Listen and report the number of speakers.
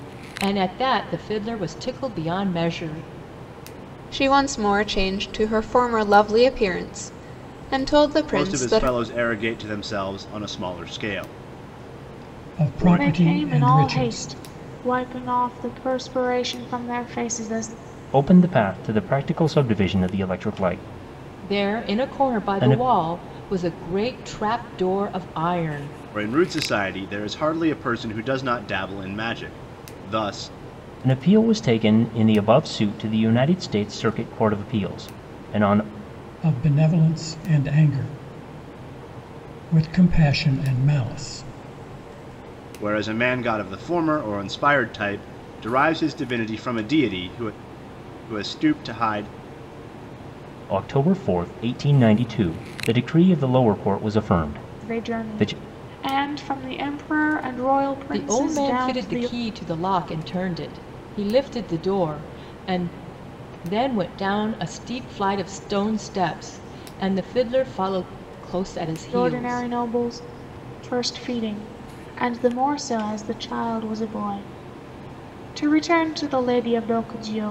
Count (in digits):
6